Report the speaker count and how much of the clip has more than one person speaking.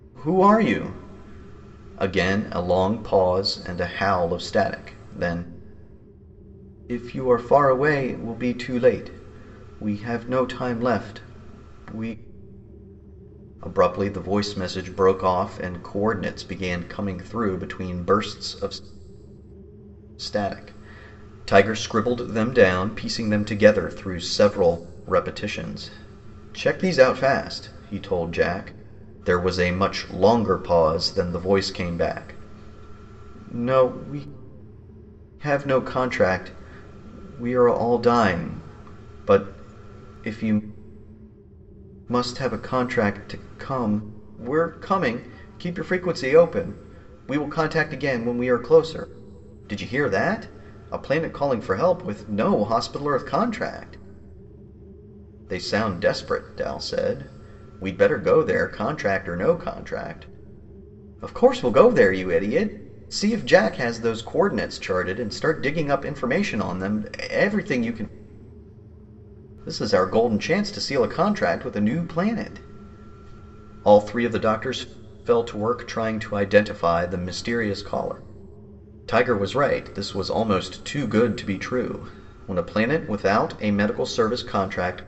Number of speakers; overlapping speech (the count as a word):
one, no overlap